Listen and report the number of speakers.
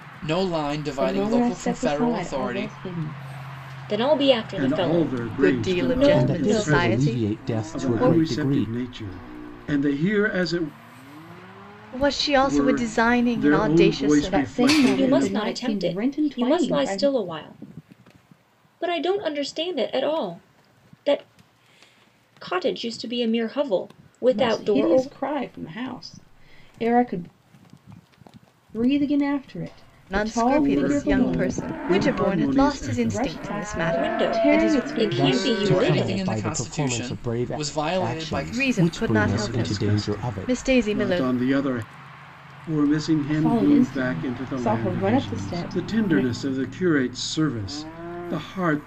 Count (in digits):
6